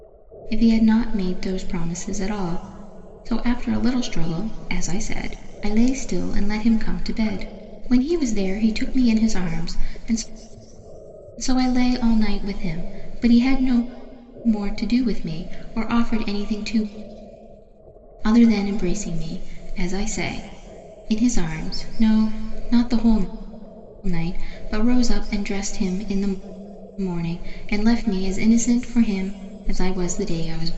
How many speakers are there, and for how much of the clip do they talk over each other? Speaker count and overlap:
1, no overlap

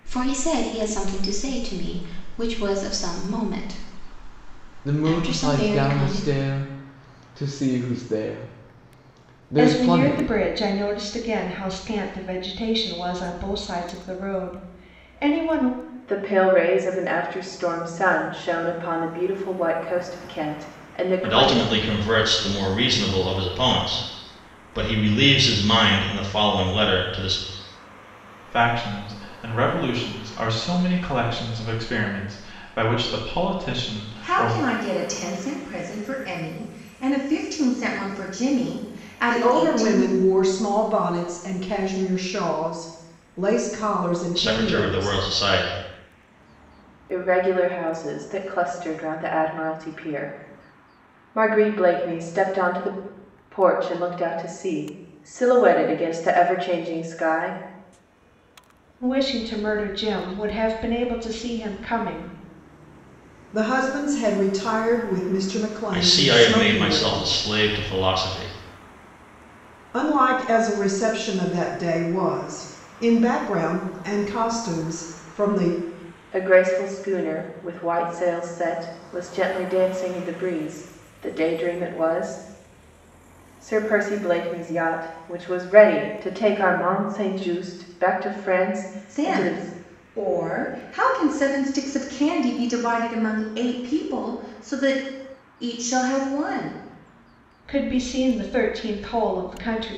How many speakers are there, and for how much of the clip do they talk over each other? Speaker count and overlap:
8, about 7%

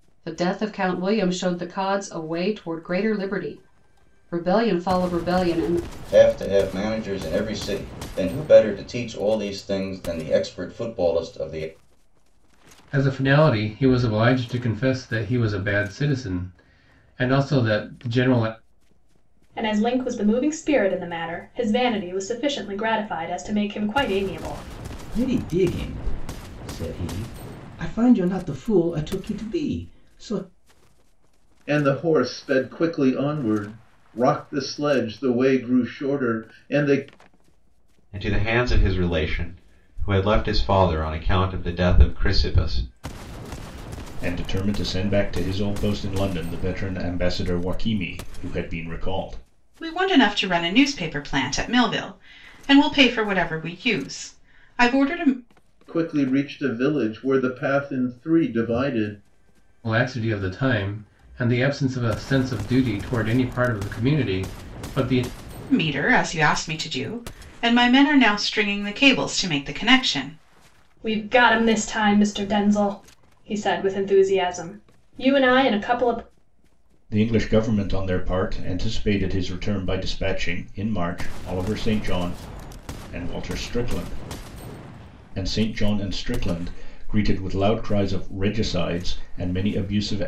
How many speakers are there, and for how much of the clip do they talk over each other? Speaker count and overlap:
9, no overlap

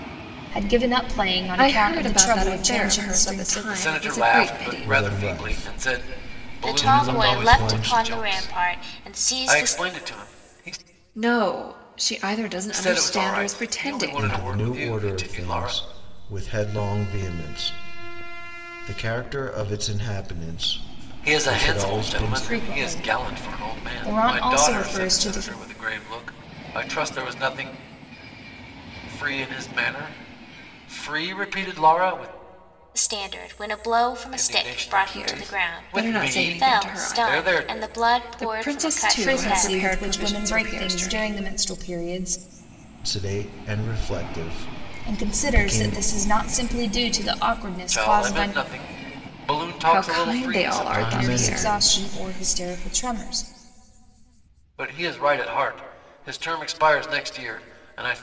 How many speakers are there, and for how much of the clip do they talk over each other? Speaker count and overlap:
5, about 46%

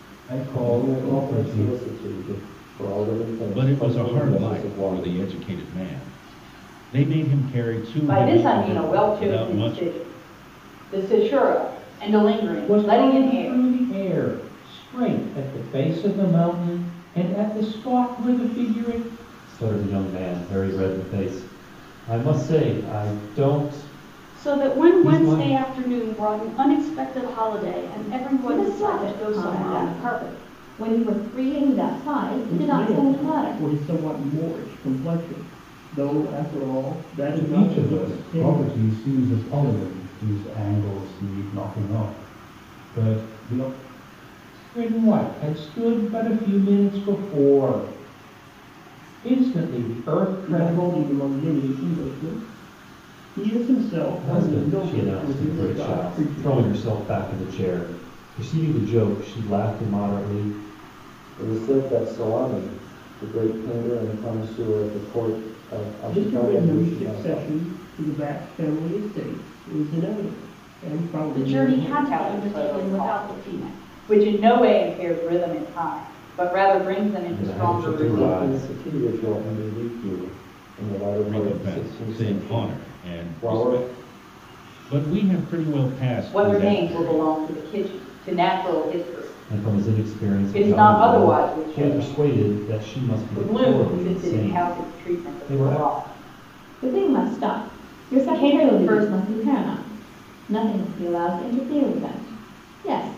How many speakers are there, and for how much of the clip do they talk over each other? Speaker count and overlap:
9, about 31%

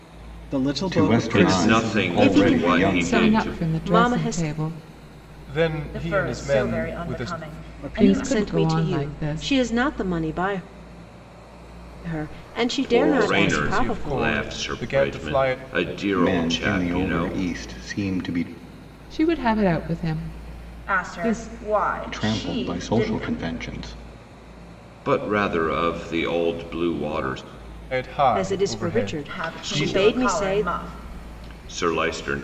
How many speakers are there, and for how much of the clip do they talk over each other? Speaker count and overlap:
7, about 48%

